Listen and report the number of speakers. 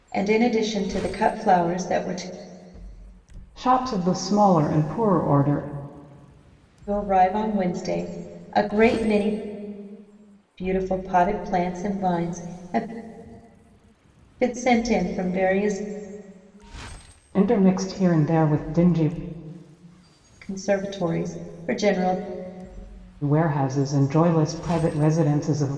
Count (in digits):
2